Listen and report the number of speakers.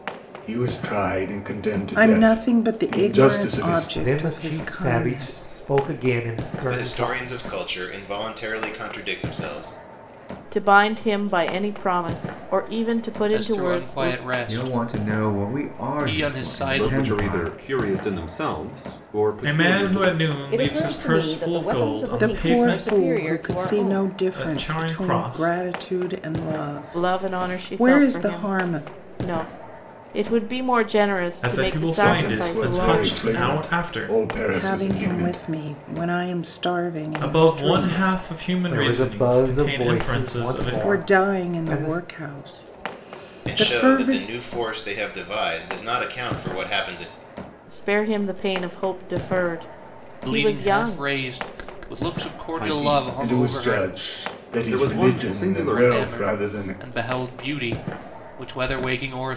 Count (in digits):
10